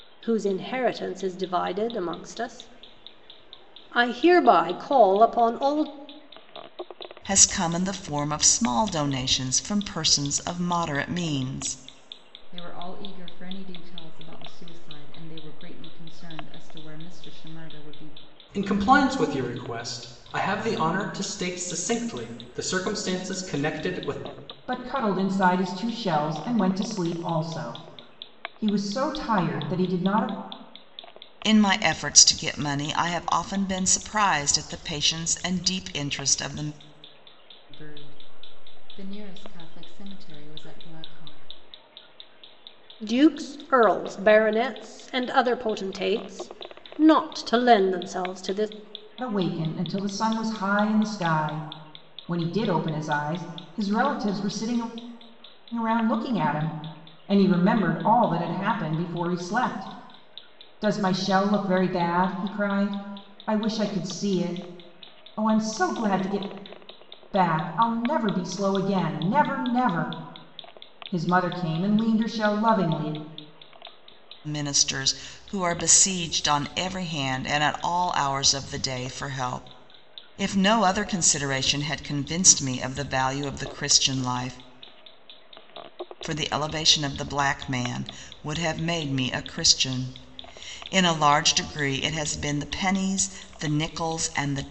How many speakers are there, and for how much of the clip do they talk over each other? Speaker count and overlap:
5, no overlap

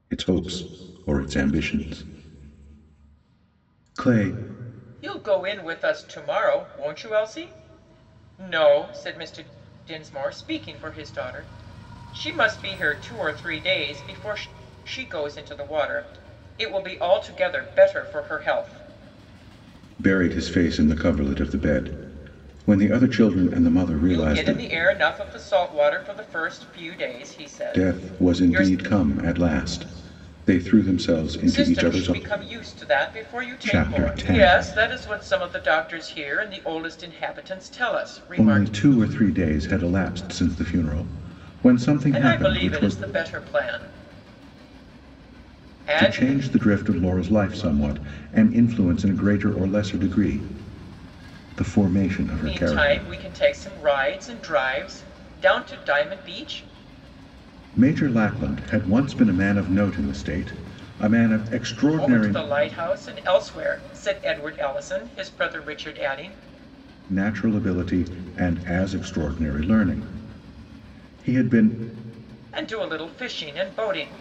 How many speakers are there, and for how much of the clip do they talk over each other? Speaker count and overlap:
2, about 9%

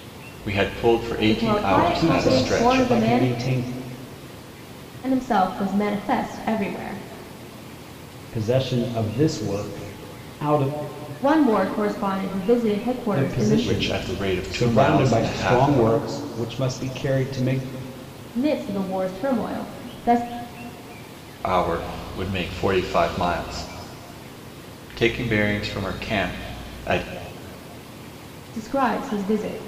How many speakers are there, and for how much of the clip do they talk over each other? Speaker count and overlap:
3, about 16%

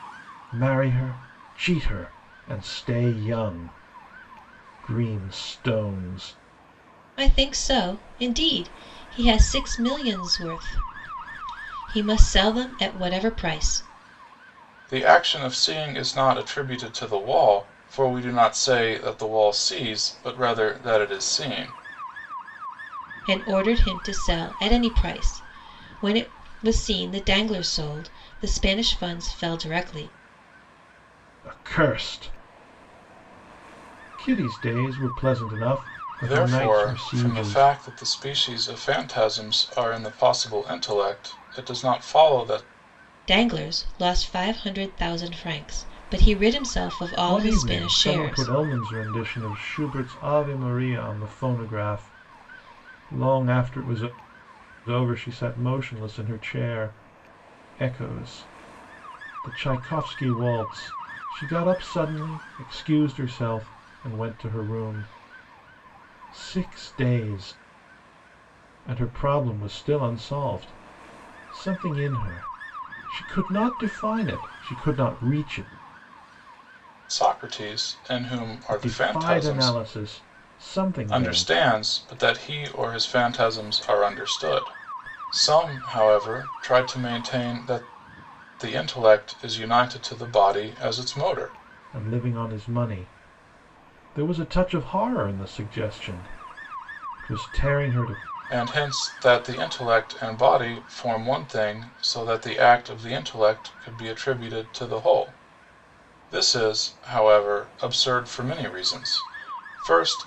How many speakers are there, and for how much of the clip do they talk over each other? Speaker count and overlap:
3, about 4%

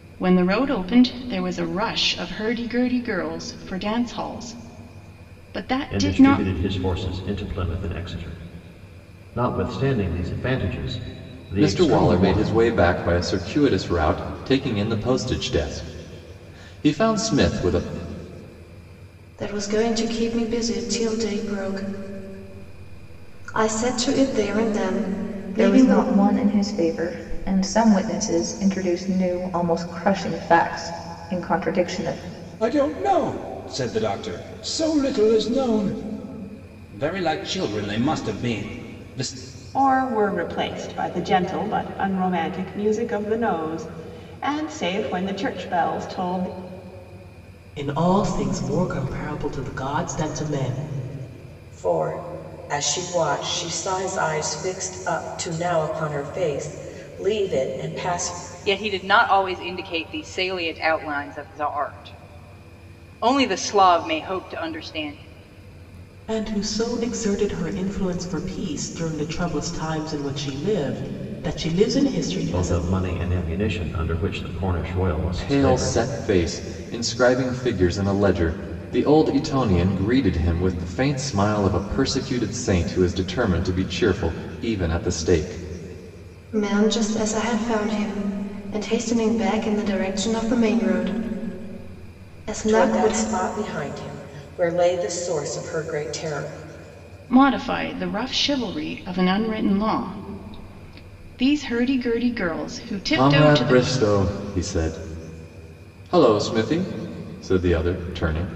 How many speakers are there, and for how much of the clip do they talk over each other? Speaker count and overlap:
10, about 4%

